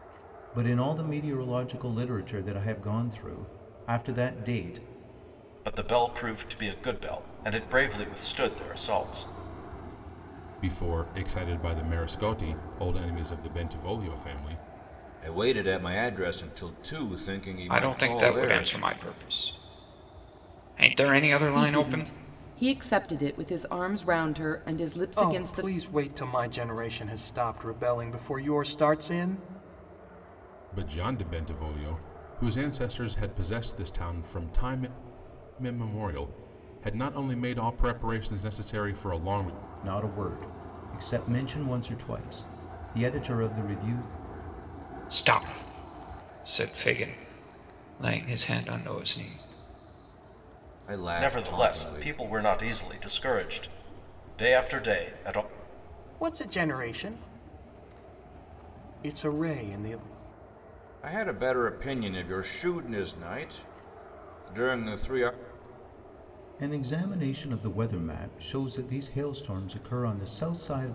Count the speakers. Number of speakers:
seven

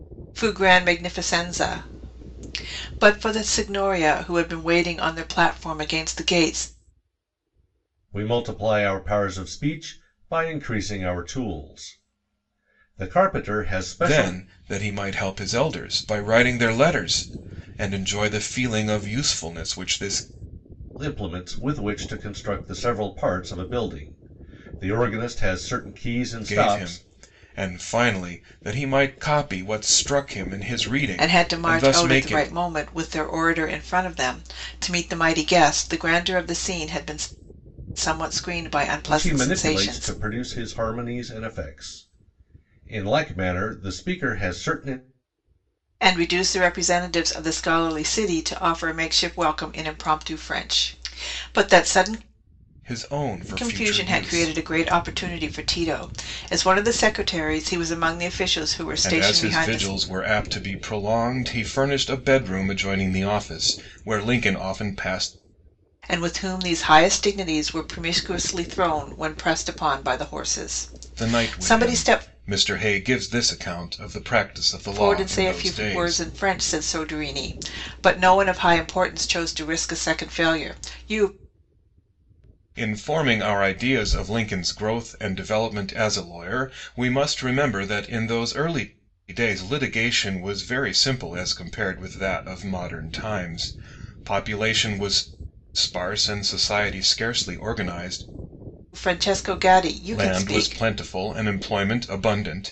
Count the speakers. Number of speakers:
three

